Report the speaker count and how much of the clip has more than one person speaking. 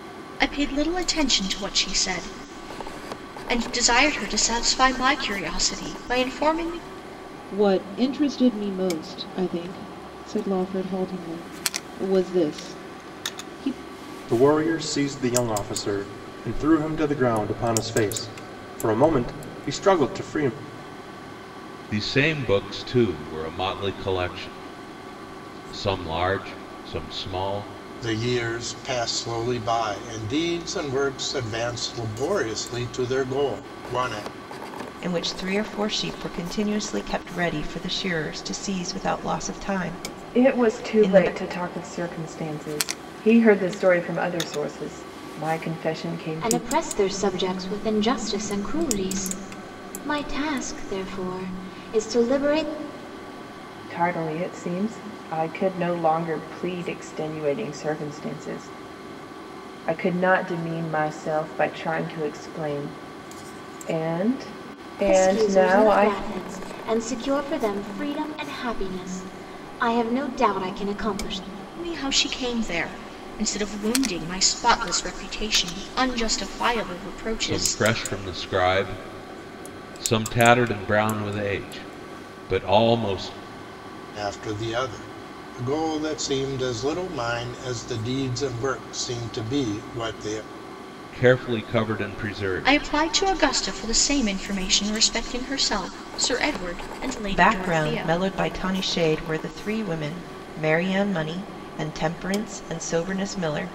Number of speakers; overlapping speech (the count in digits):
8, about 4%